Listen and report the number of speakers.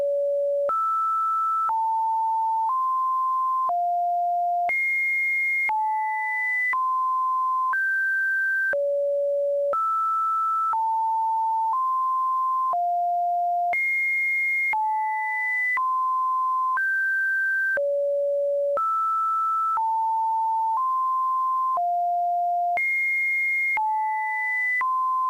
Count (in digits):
0